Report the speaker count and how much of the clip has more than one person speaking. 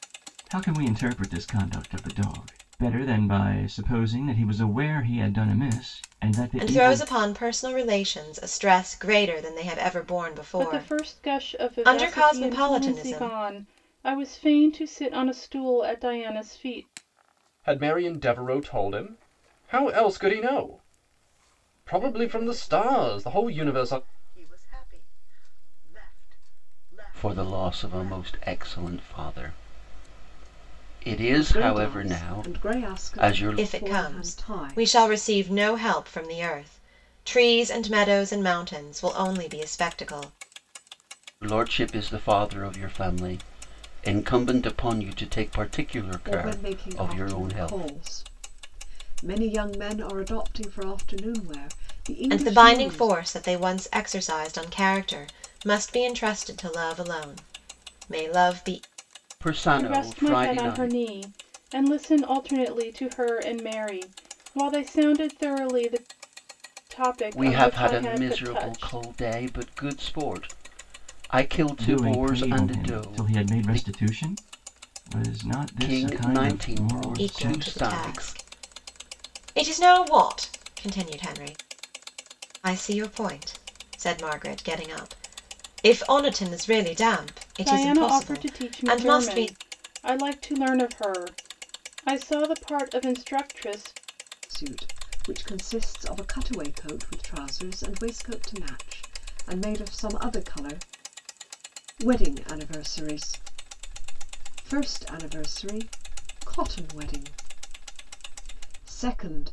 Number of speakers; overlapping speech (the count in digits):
7, about 21%